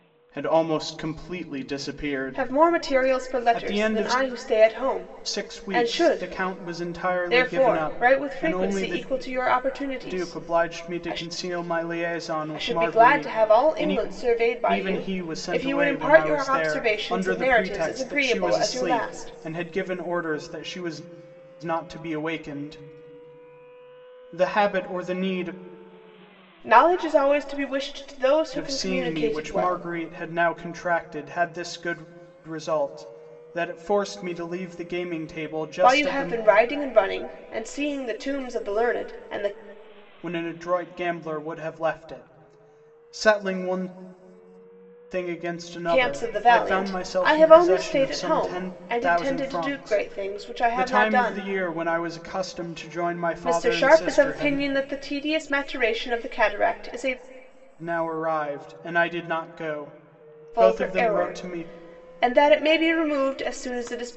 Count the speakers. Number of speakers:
2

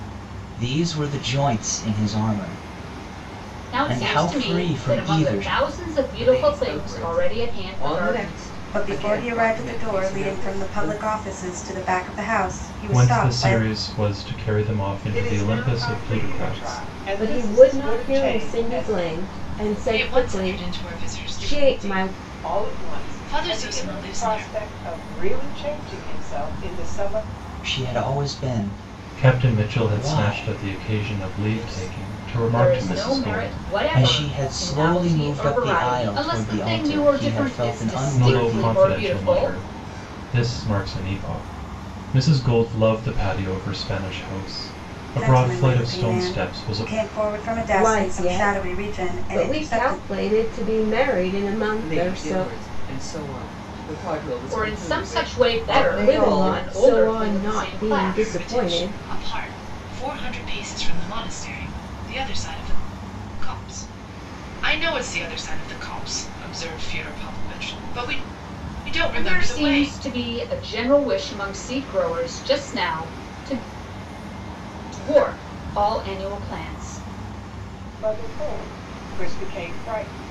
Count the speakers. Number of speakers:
8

